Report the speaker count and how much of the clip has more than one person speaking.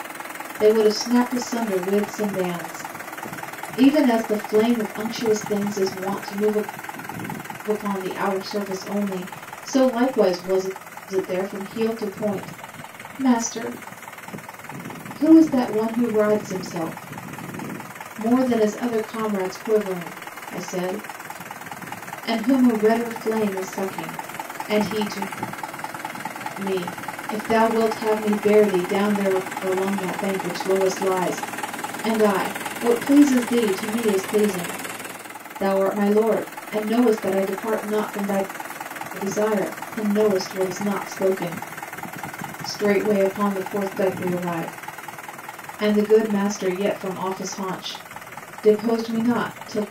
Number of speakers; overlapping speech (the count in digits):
1, no overlap